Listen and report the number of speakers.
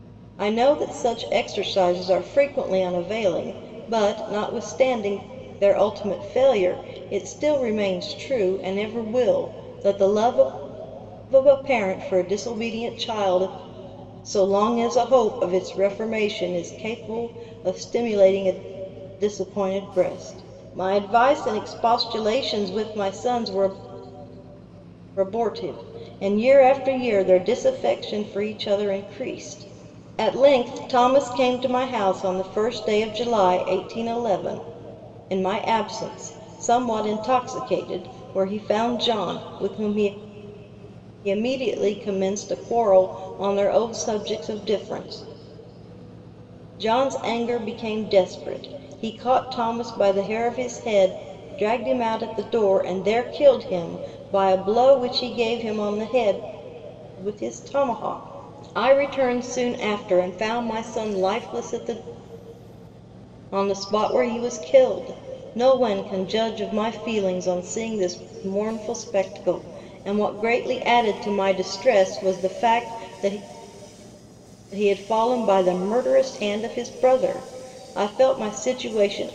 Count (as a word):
one